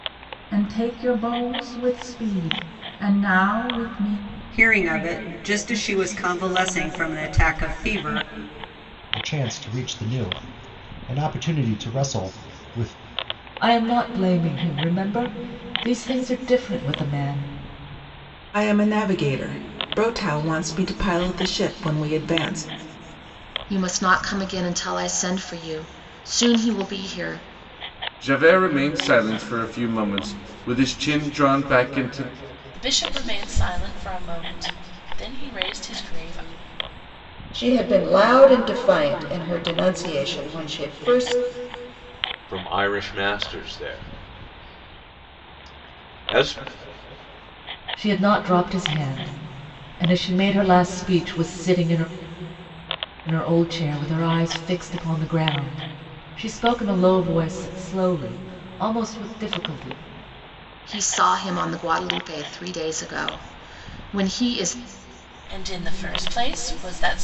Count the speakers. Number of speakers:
ten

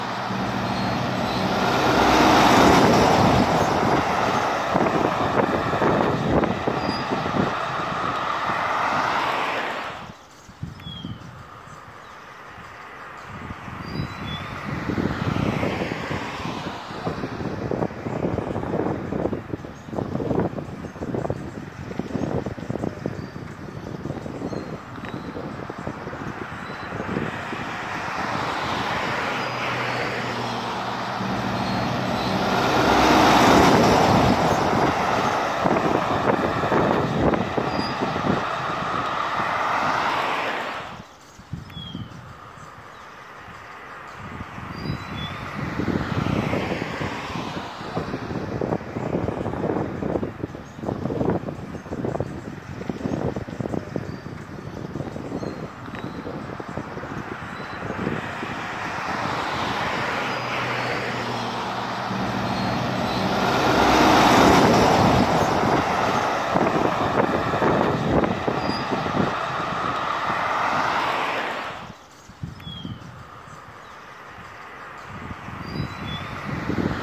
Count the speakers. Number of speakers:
zero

